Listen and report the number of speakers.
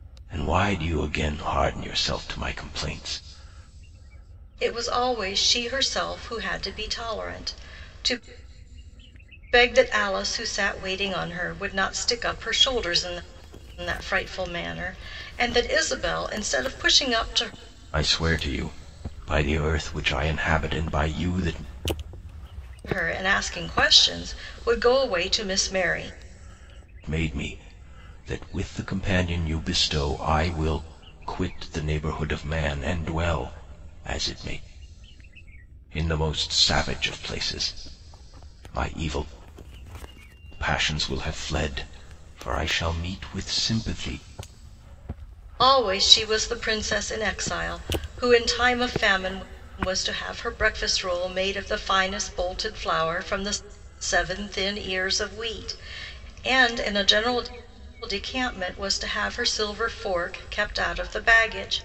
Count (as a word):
two